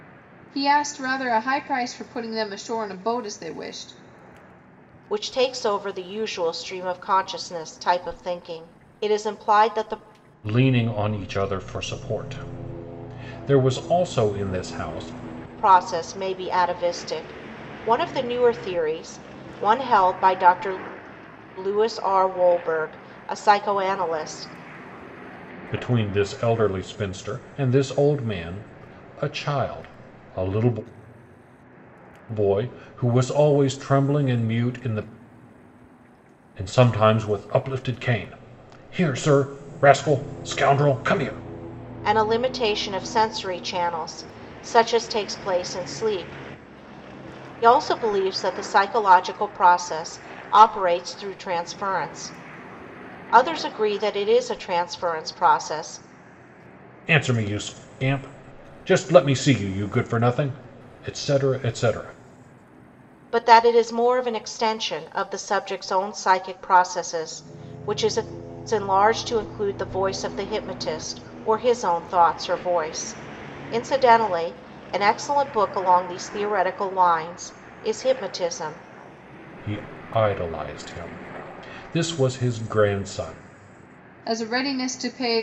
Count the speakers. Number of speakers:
3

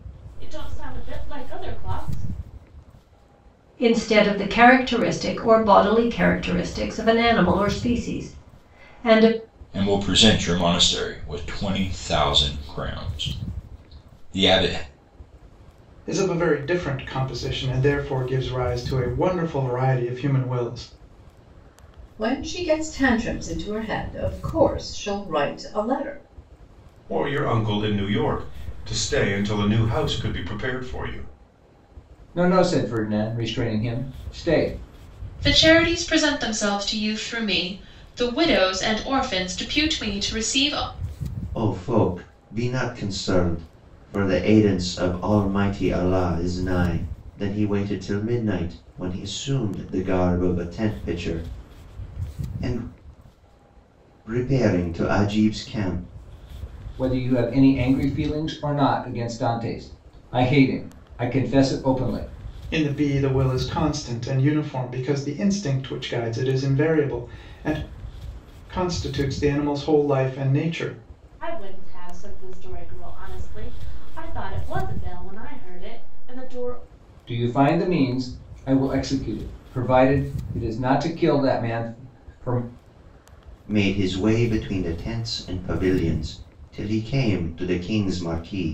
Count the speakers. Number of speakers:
9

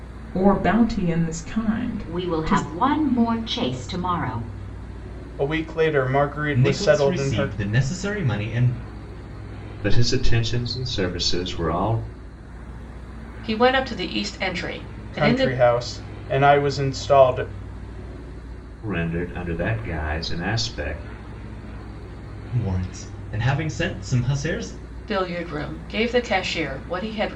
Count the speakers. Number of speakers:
6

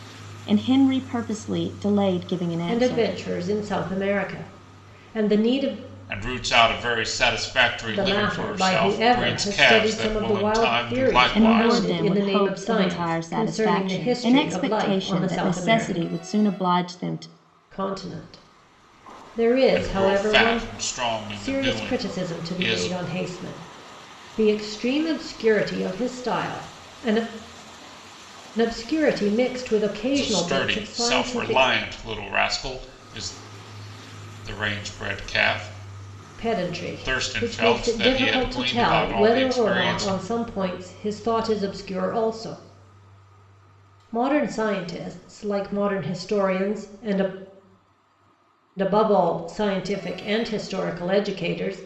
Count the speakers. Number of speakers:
3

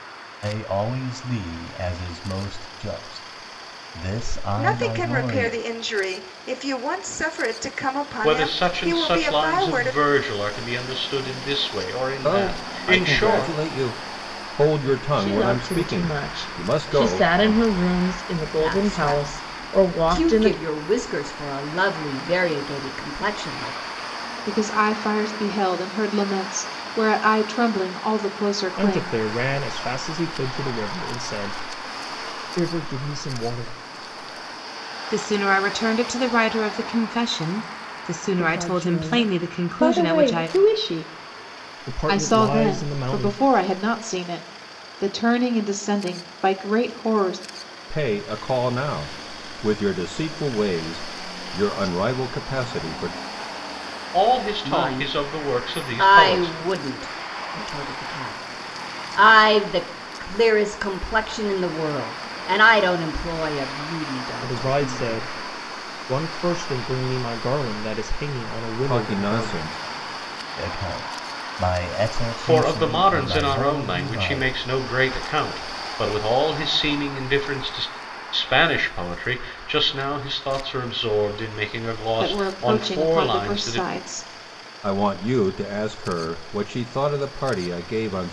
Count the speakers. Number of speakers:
10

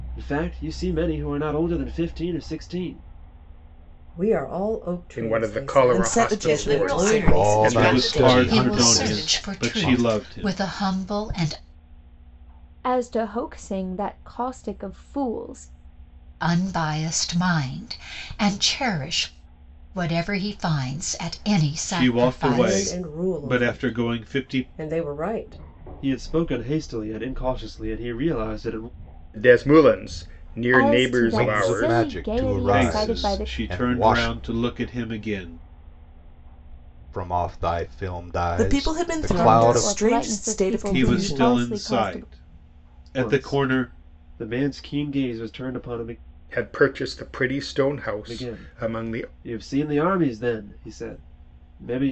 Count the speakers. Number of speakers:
9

